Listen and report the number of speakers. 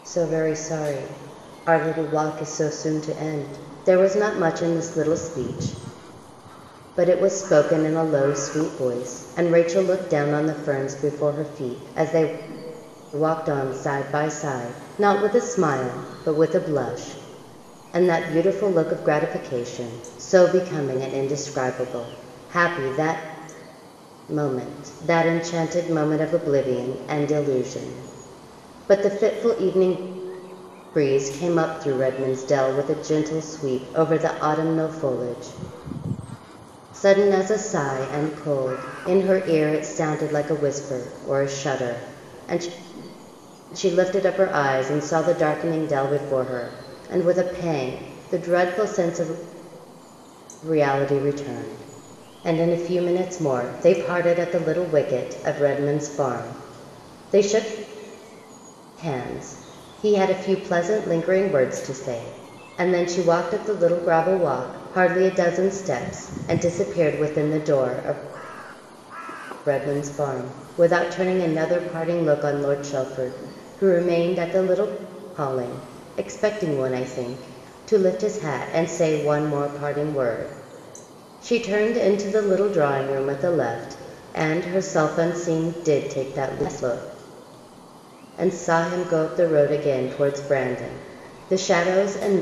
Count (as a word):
one